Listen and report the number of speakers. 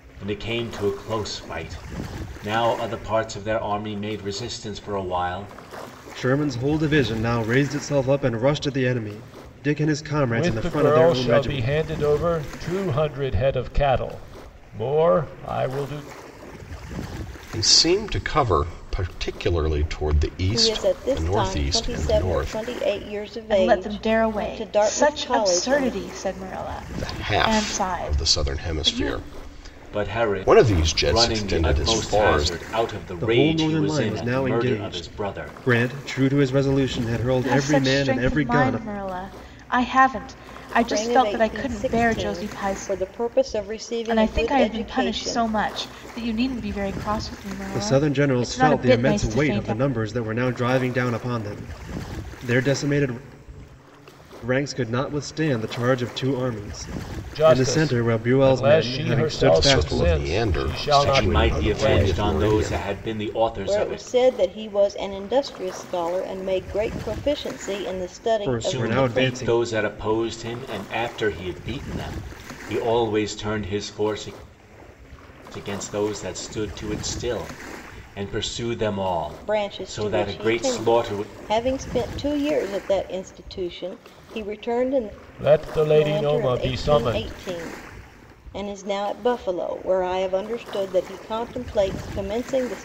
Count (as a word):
six